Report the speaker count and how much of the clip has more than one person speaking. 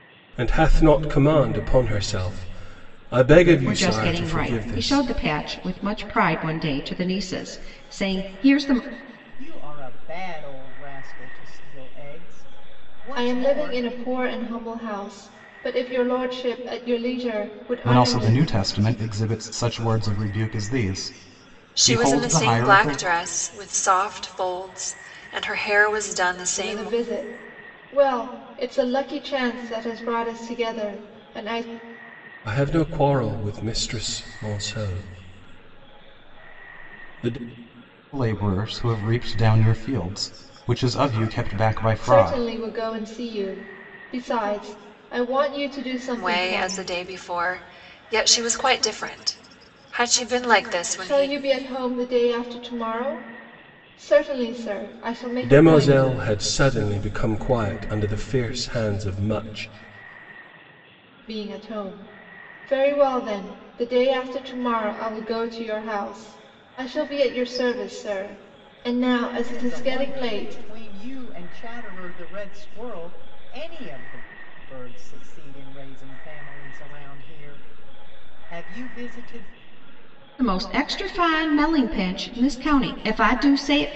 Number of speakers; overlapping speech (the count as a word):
six, about 9%